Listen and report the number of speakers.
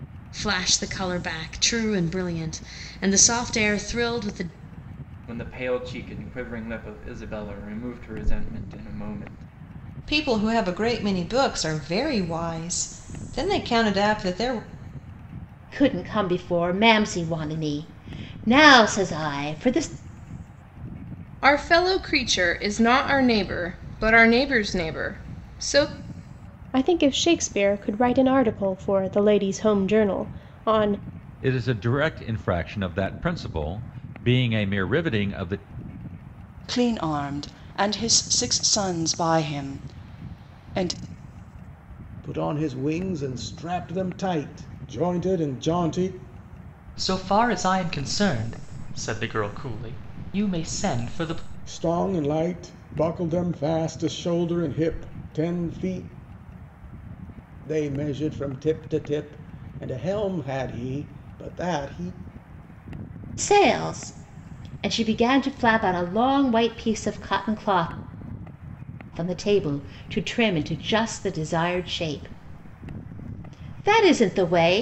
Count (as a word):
ten